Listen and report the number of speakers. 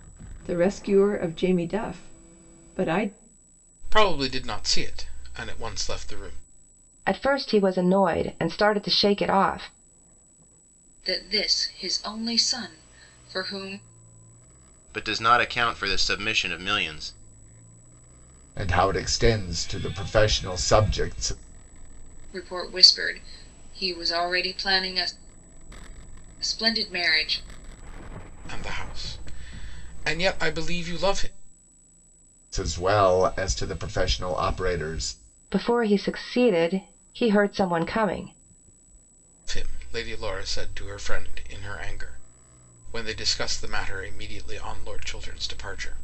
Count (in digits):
6